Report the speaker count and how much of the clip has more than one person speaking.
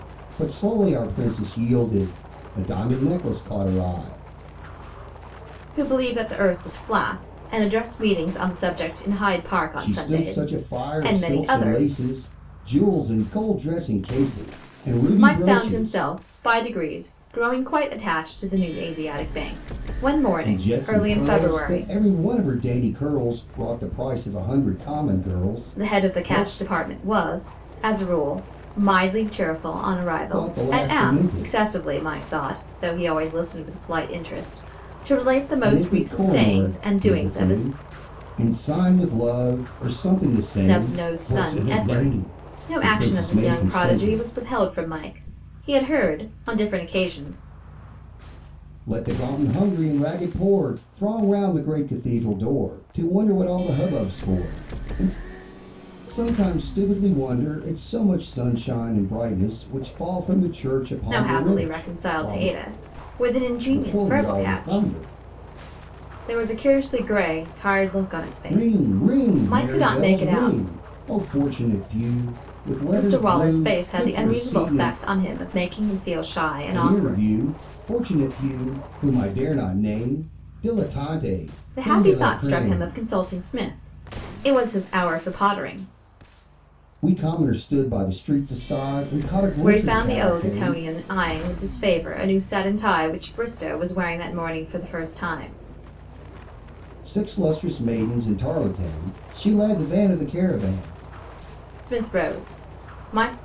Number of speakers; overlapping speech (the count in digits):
2, about 22%